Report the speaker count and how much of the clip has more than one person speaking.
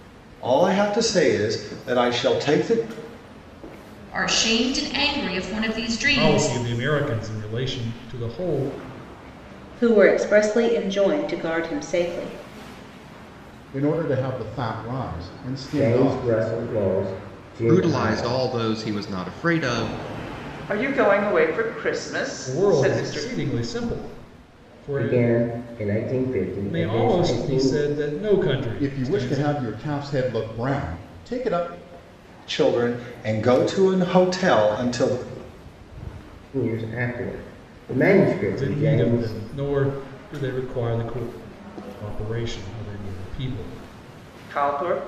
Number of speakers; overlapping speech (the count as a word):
eight, about 13%